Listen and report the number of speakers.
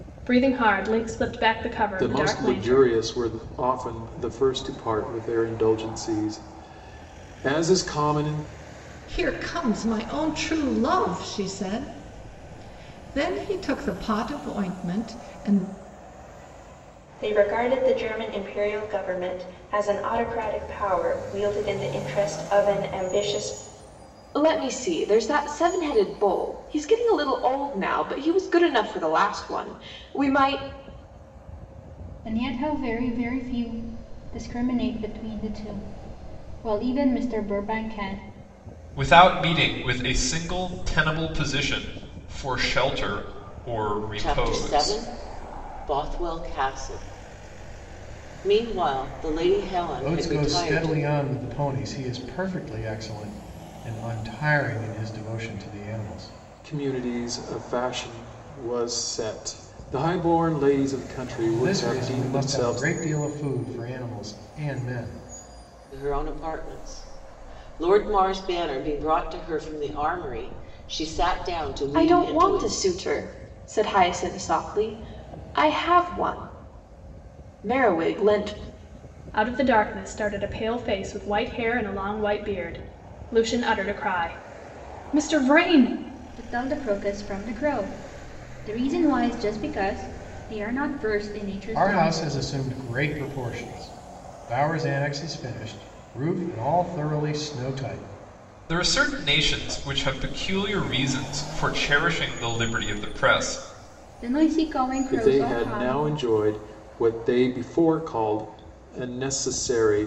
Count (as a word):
nine